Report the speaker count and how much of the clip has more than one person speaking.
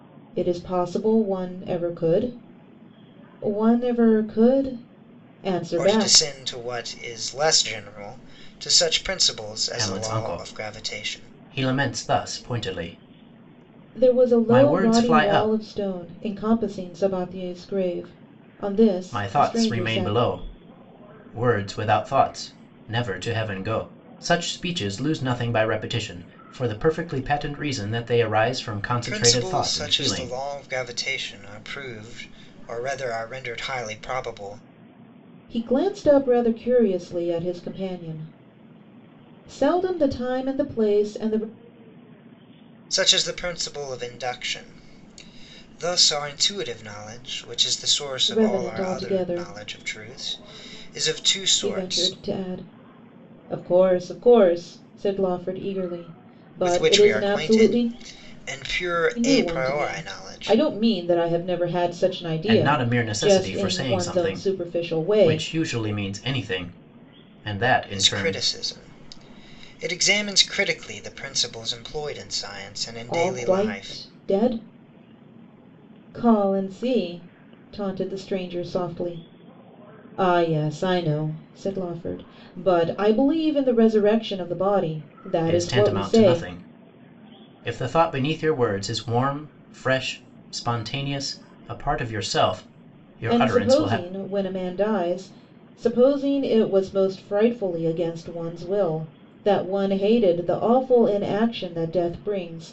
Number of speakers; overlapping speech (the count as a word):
three, about 17%